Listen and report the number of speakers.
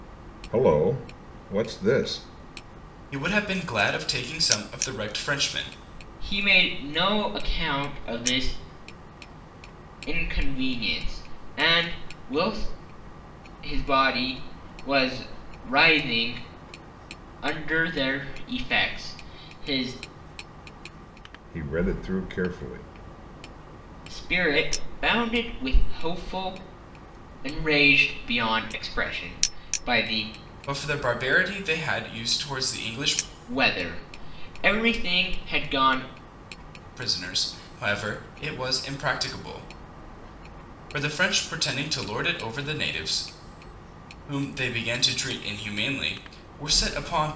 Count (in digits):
3